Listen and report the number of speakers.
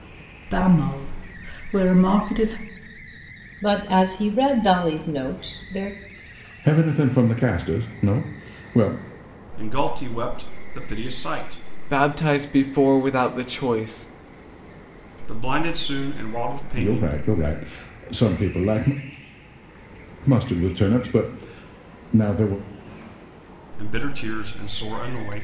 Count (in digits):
5